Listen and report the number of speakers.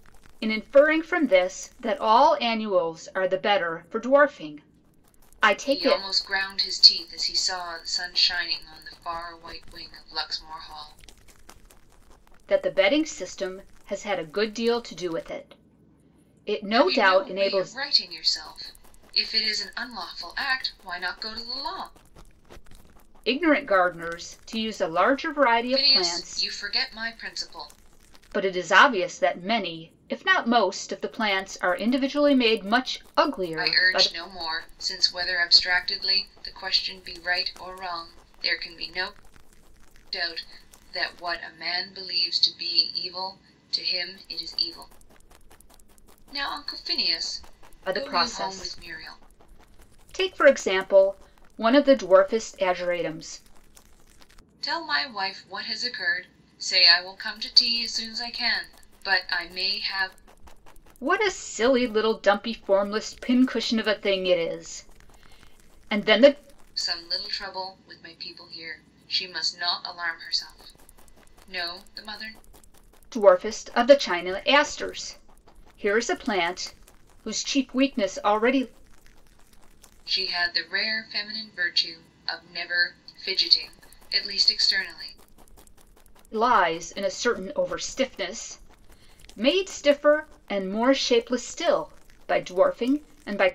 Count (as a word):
two